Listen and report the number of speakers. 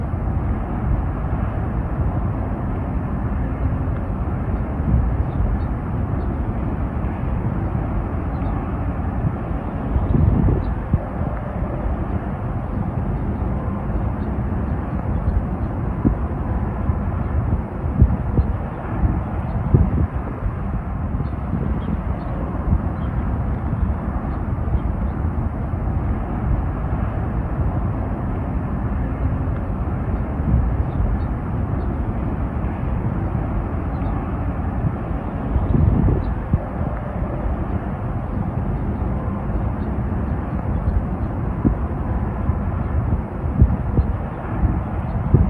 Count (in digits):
0